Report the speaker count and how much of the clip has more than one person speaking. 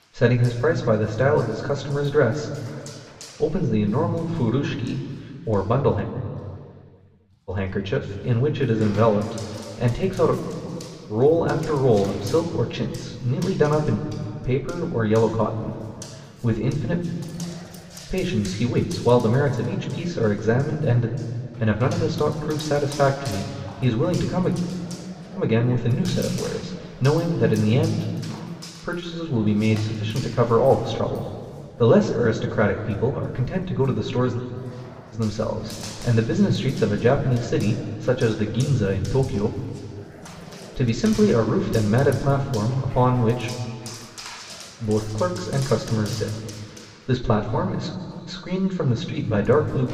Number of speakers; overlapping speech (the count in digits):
1, no overlap